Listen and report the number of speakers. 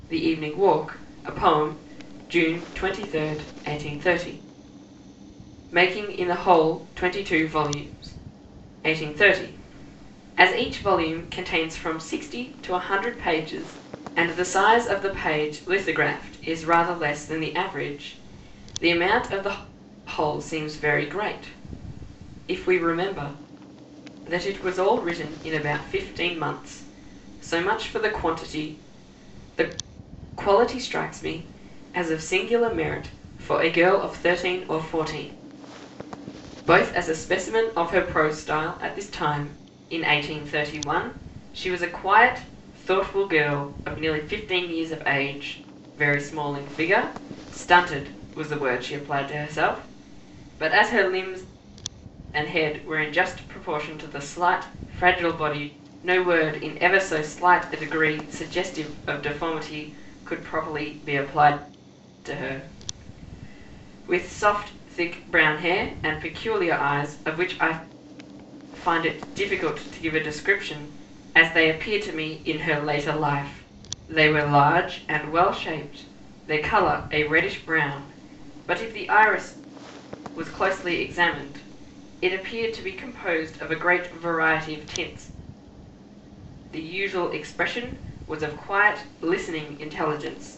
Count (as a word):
one